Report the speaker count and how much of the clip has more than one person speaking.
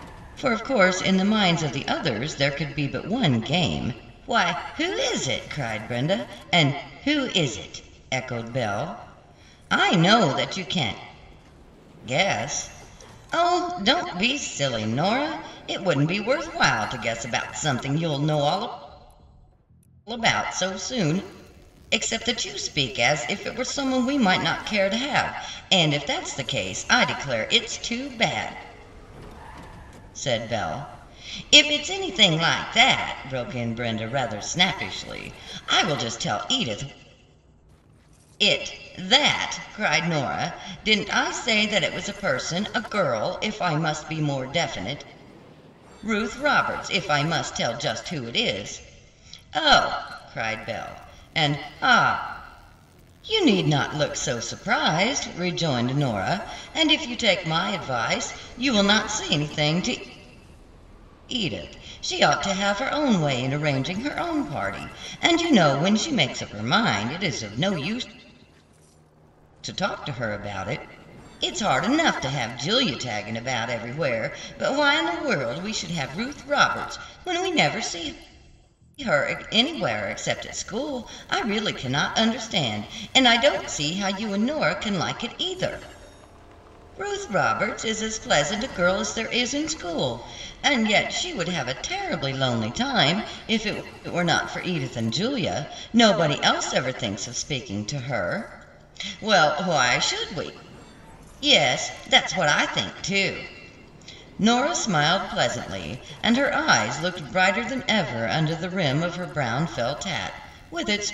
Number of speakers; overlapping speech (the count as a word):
one, no overlap